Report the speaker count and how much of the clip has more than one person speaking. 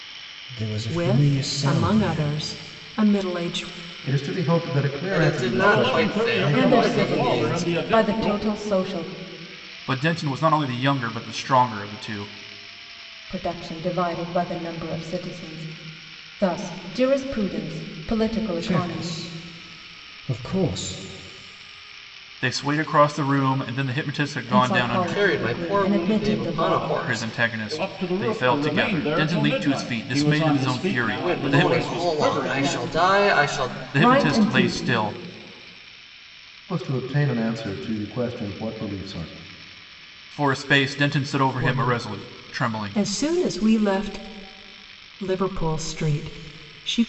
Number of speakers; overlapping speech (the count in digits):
7, about 37%